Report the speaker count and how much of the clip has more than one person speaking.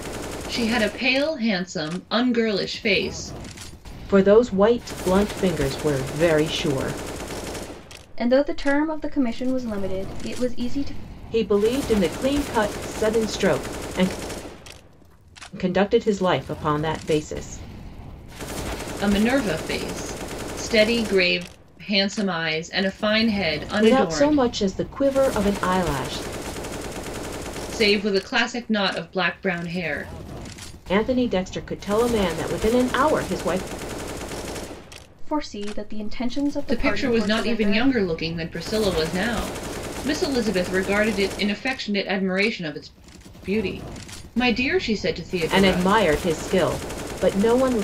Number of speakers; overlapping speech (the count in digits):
3, about 5%